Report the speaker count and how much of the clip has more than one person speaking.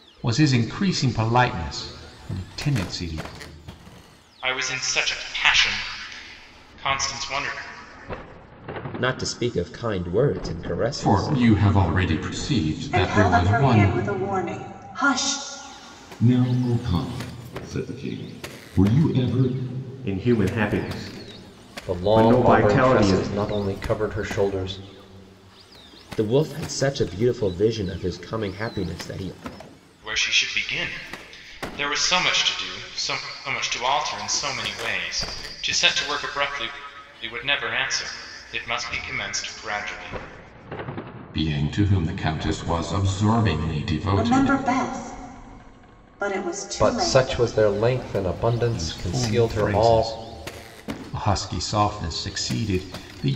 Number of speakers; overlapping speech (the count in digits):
8, about 10%